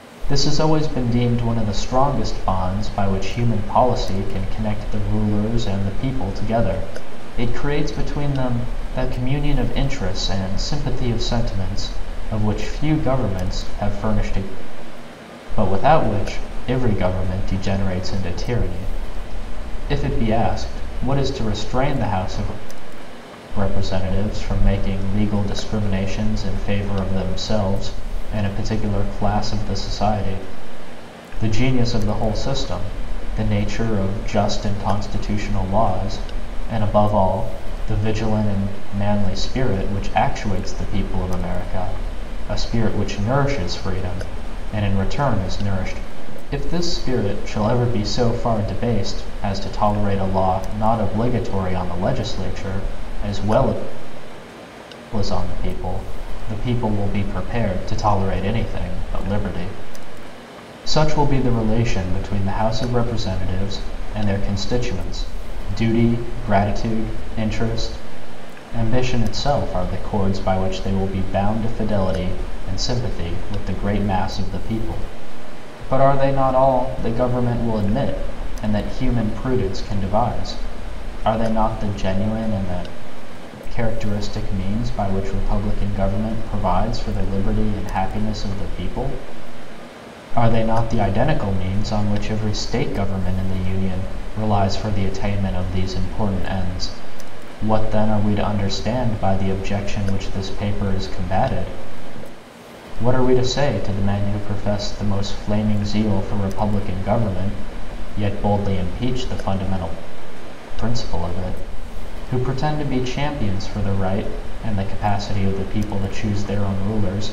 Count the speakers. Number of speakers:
one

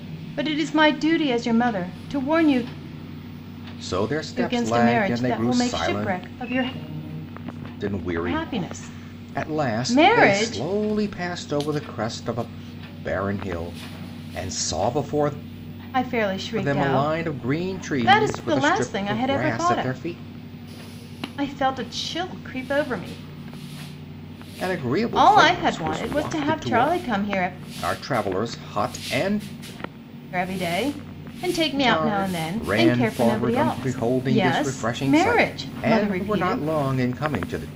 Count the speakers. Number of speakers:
two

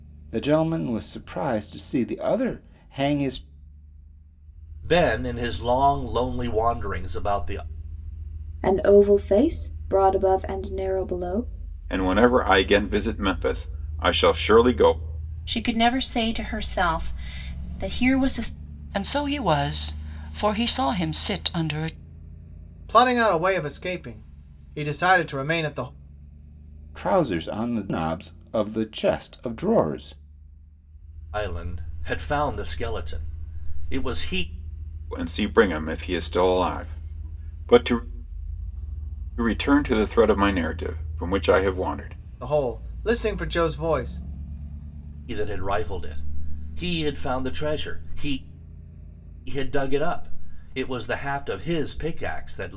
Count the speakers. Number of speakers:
seven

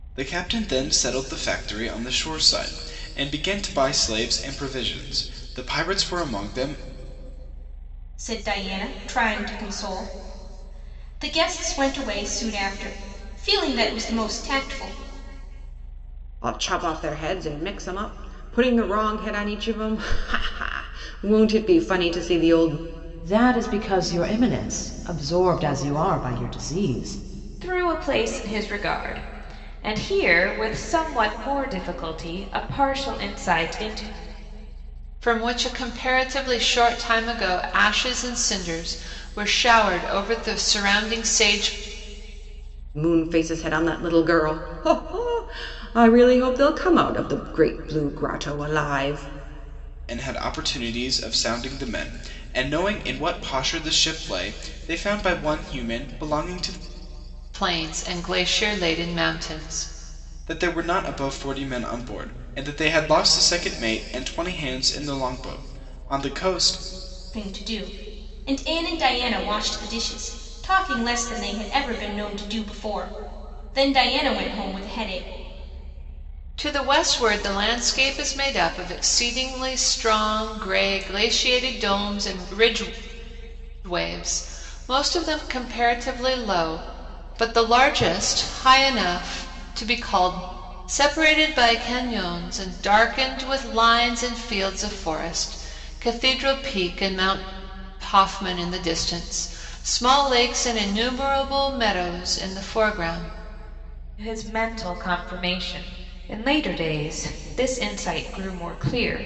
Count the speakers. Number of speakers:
six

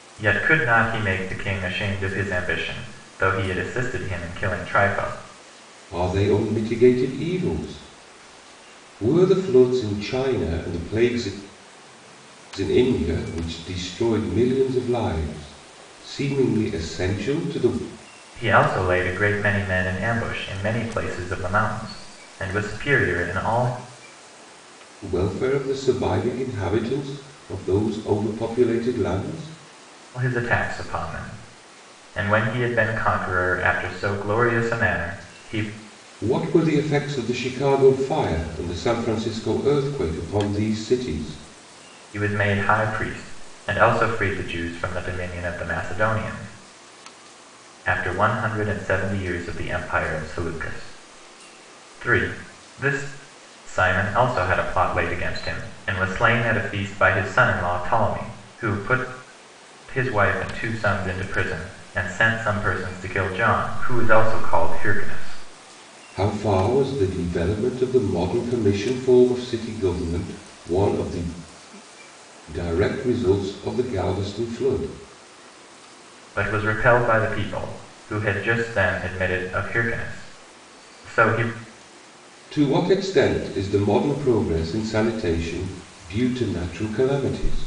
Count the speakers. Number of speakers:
two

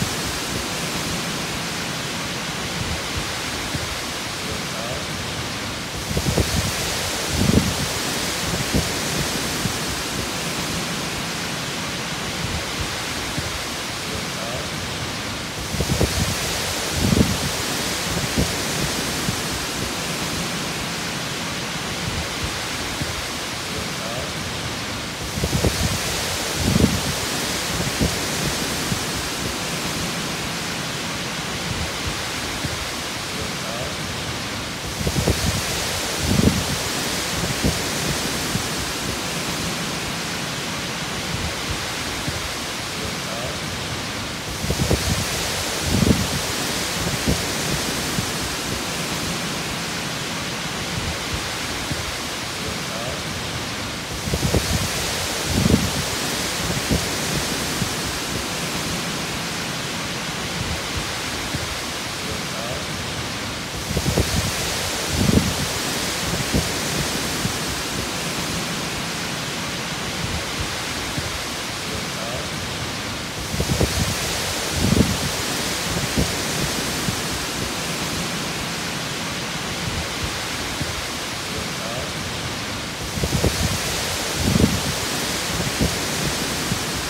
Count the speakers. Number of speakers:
zero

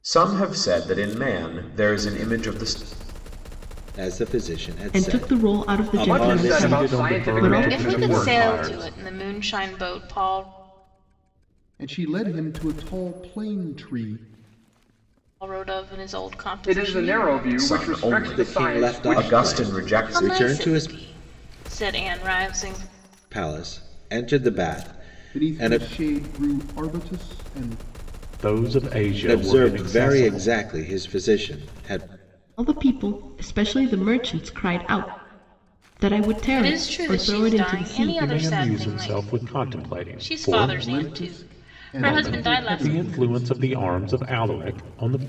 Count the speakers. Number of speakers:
seven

